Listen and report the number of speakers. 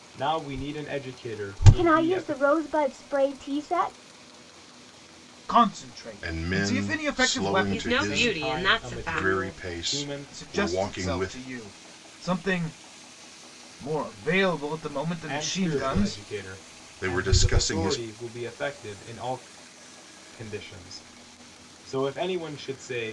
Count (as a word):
five